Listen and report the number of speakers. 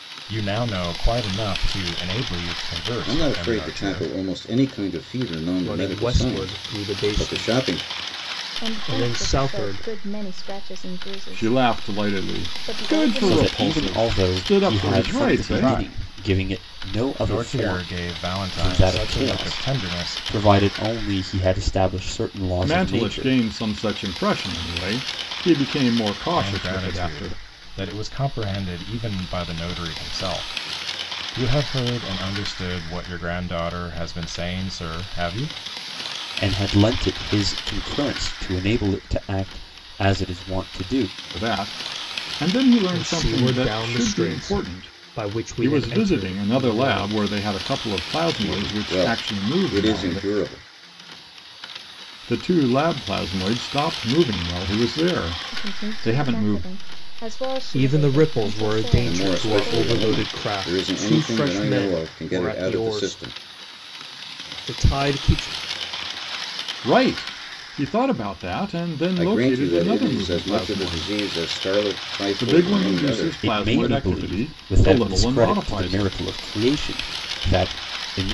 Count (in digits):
6